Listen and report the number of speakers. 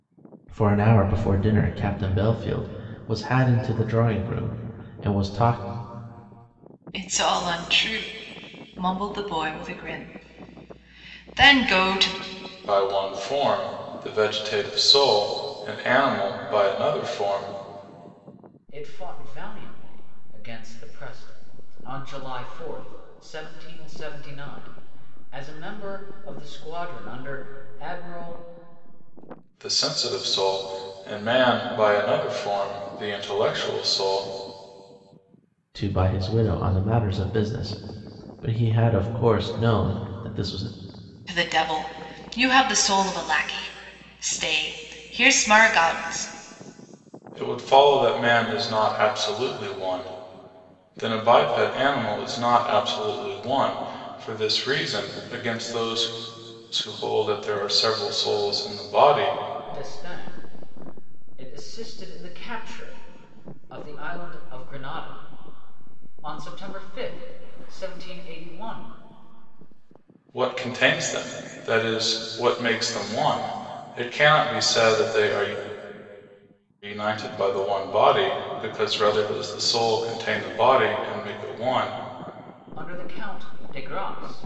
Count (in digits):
4